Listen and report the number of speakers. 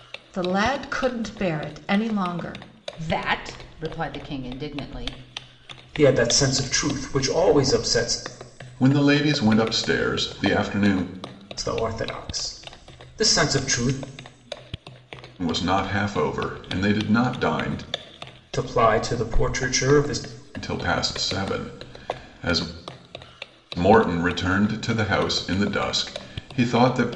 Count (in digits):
4